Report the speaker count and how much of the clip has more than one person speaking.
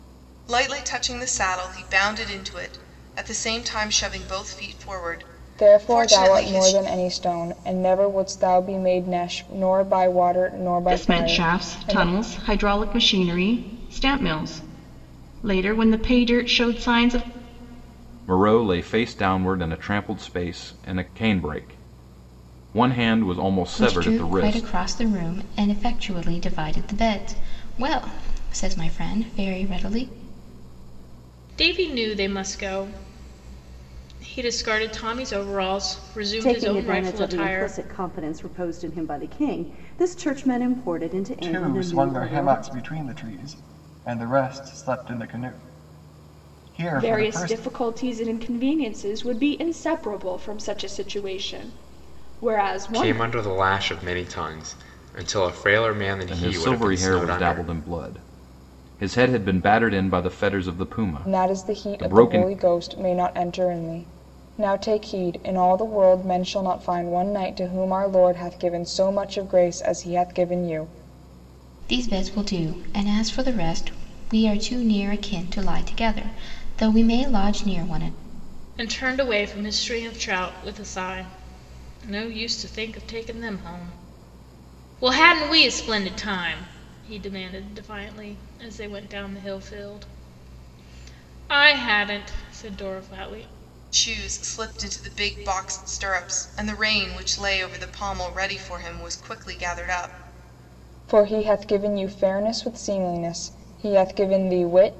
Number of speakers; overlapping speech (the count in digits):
10, about 9%